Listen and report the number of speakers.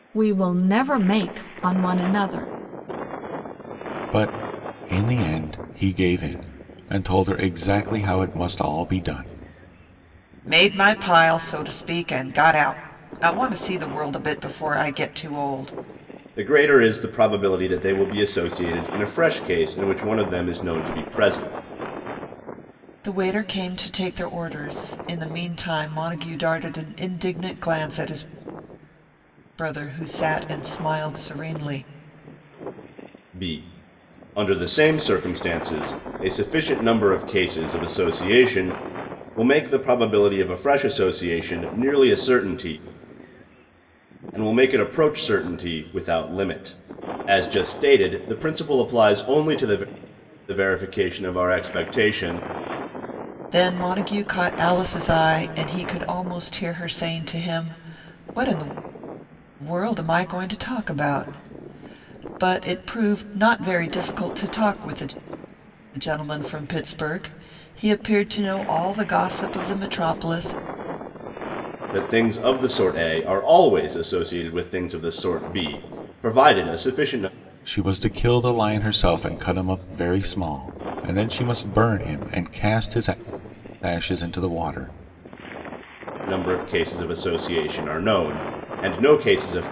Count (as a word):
four